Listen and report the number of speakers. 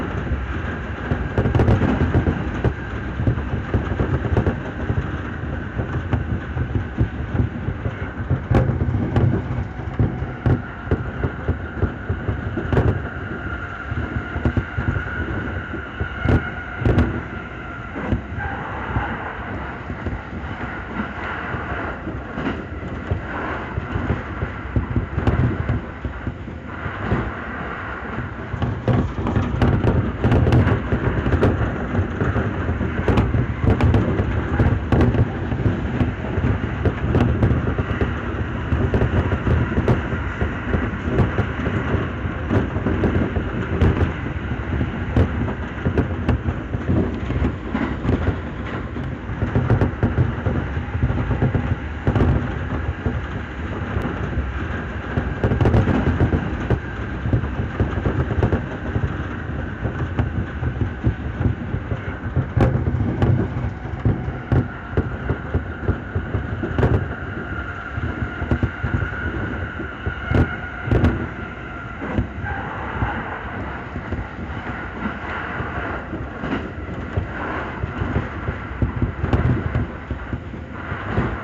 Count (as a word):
zero